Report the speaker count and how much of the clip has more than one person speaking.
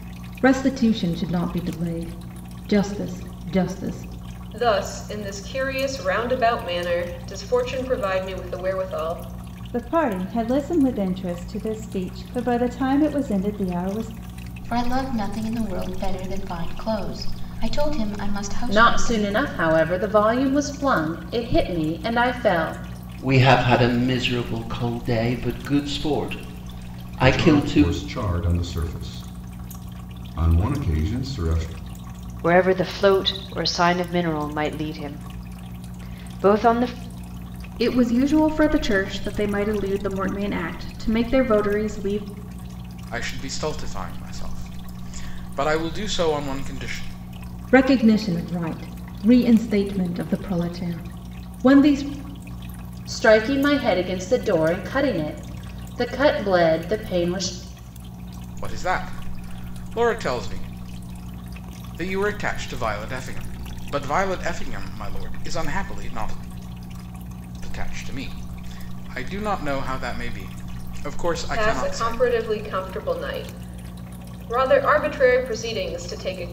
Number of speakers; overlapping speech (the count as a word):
ten, about 3%